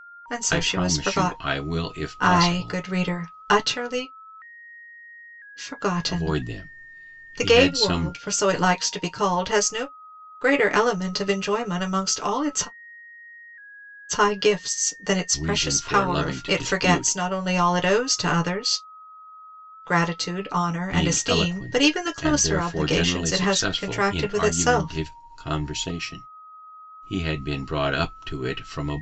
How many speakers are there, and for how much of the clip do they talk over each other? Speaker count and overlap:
2, about 33%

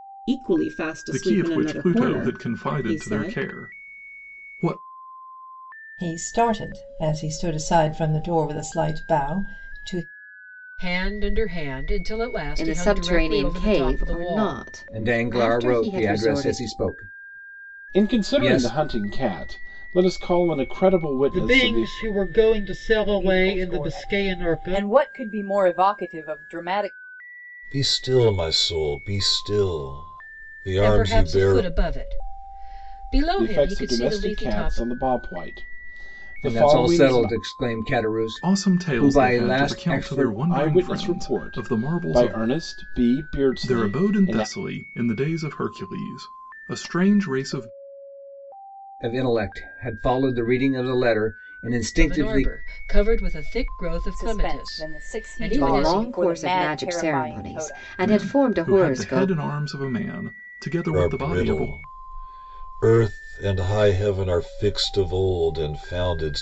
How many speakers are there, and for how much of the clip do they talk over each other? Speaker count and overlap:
10, about 36%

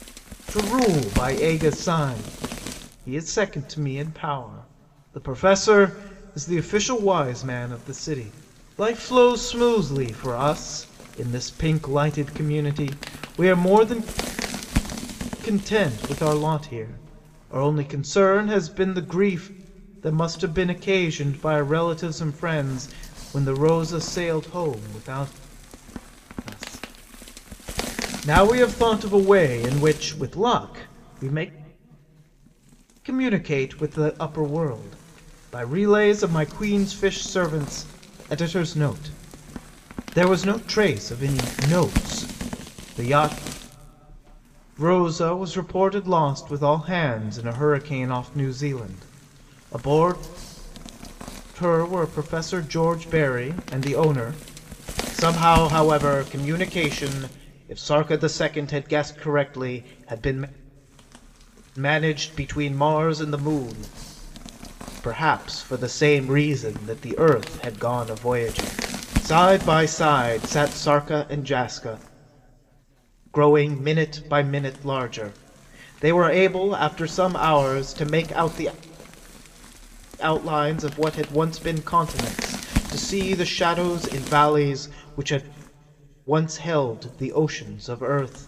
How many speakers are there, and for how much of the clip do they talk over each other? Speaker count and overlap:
1, no overlap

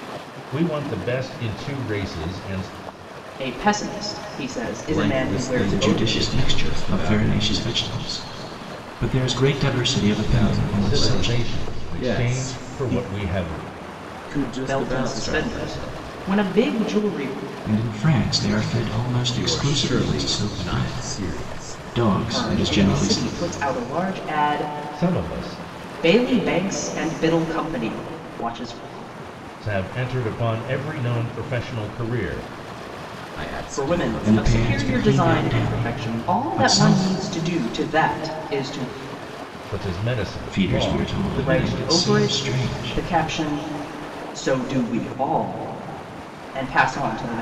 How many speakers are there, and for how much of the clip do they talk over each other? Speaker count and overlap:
4, about 38%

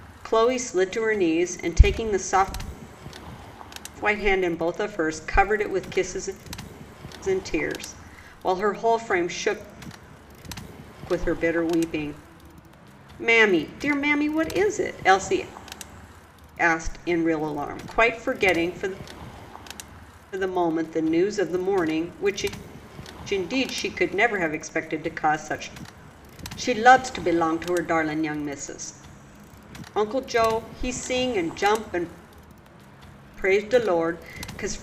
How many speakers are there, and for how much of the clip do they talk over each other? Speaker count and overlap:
1, no overlap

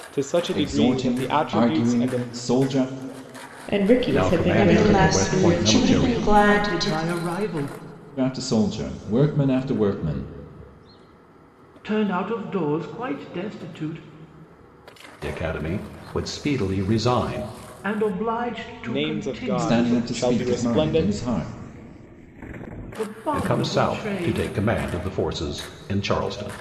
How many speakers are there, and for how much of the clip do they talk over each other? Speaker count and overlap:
6, about 31%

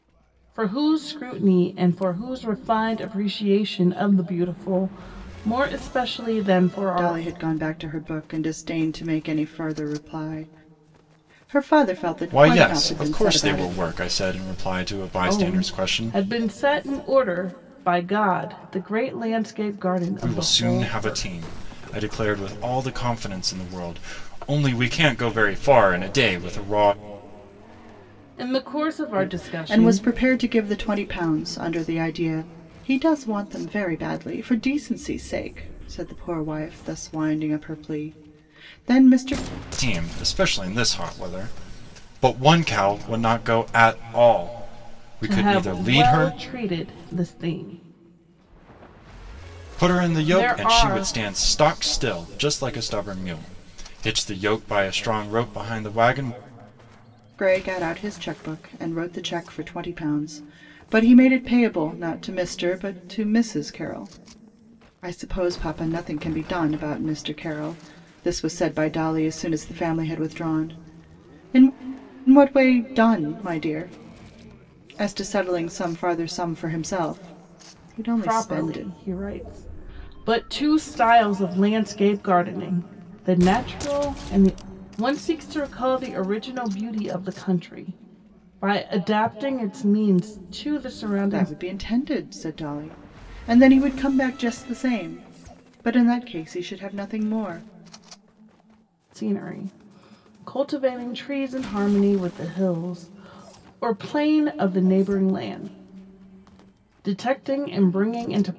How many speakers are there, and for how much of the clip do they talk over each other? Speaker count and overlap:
3, about 8%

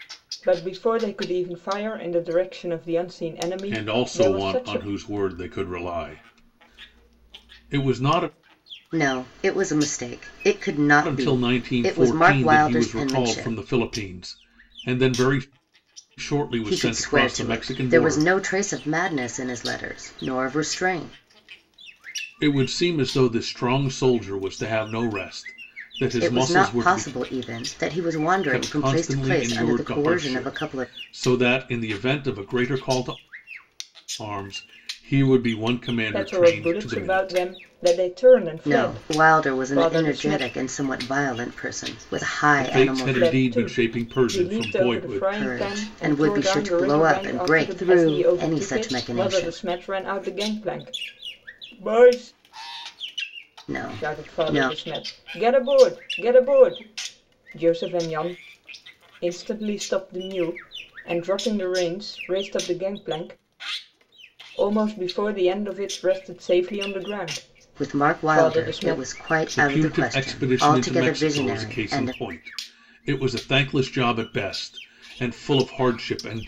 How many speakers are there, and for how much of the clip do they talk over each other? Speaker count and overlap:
3, about 32%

